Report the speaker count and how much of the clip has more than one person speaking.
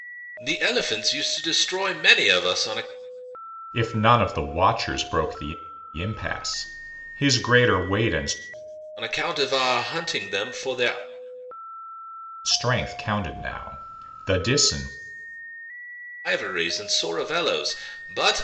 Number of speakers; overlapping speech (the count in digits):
2, no overlap